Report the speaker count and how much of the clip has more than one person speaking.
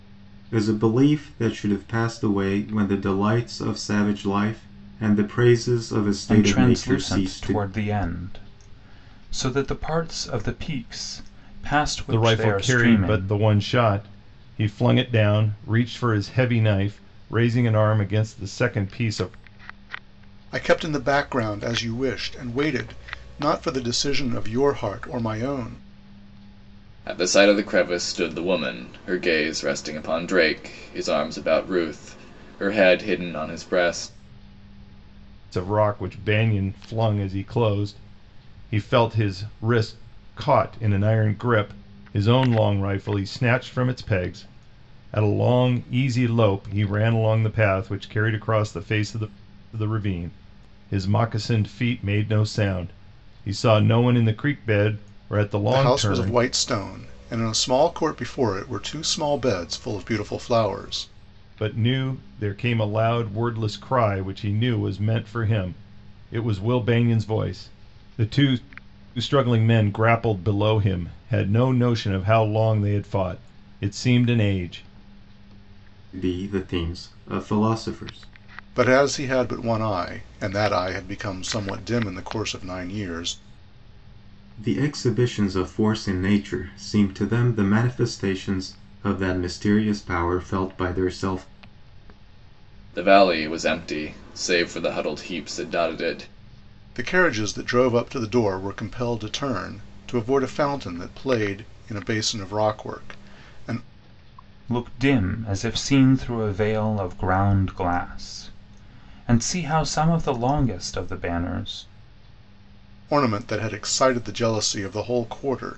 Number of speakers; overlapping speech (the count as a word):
five, about 3%